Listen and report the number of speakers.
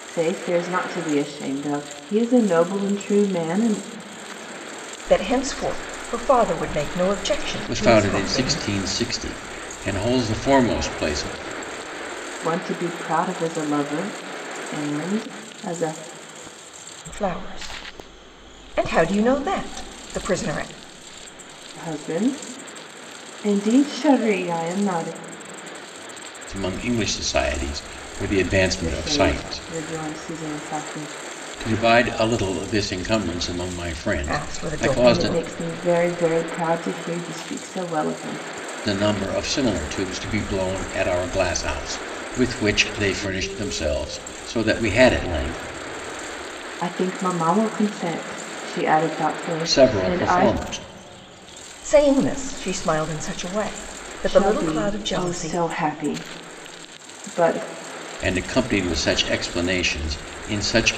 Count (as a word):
three